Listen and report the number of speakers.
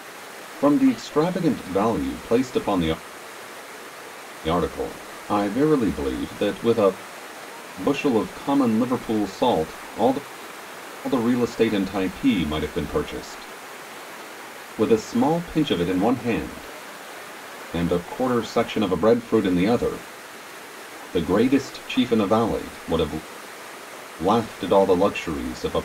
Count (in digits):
1